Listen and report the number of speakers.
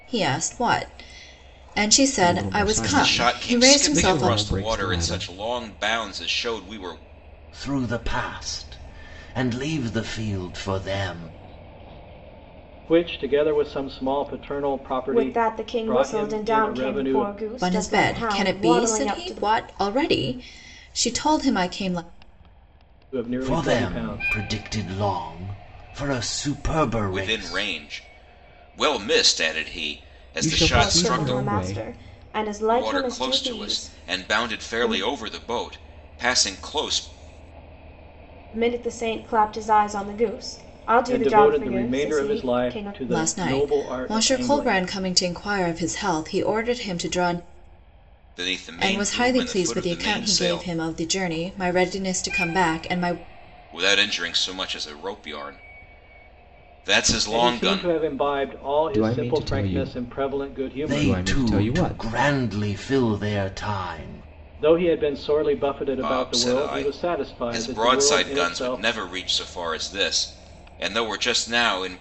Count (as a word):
six